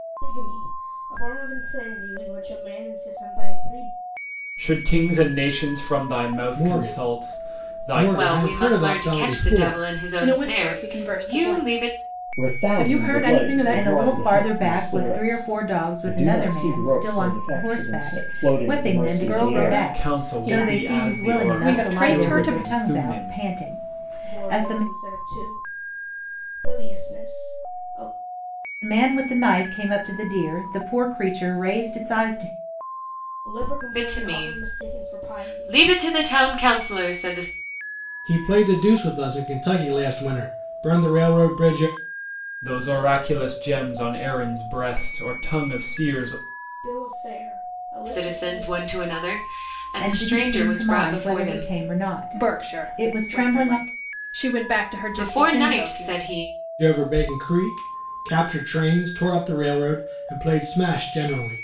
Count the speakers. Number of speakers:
seven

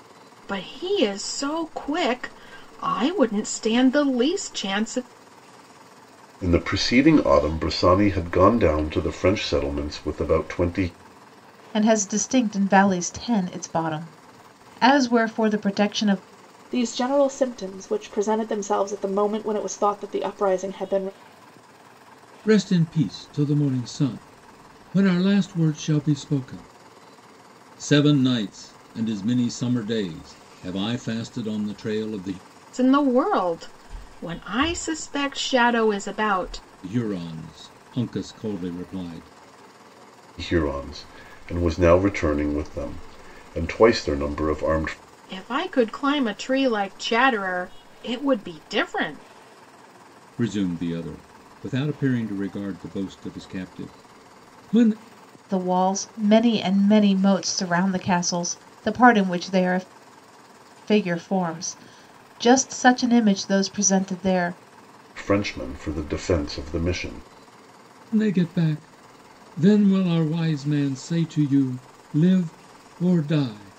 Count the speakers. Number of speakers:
five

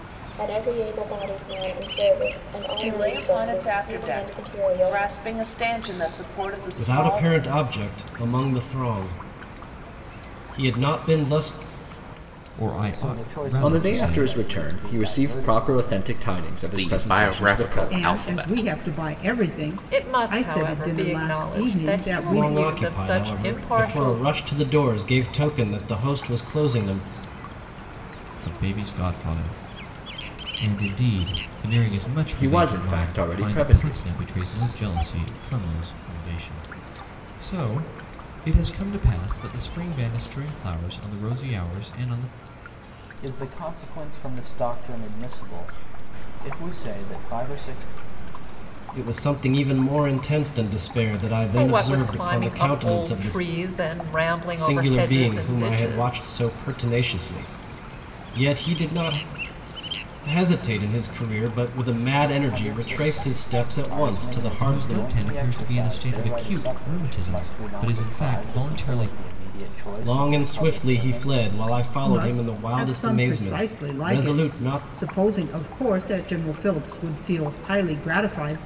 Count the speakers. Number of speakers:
nine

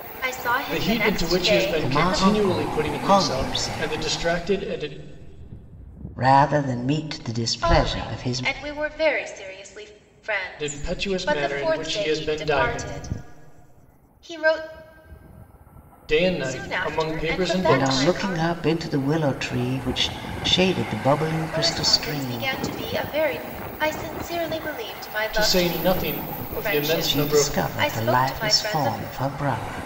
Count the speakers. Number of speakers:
three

